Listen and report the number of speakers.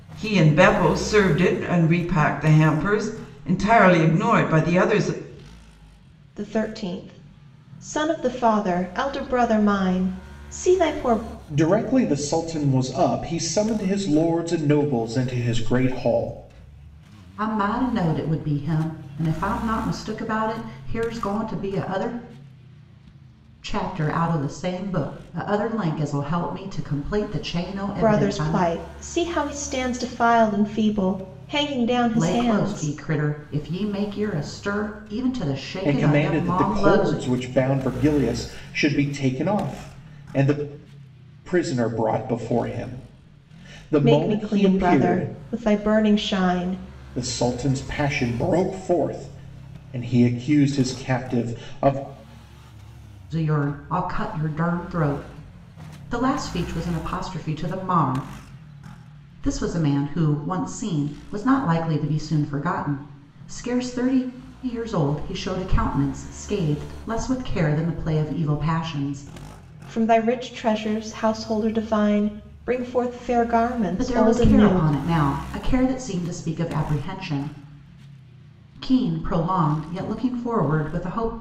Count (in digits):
4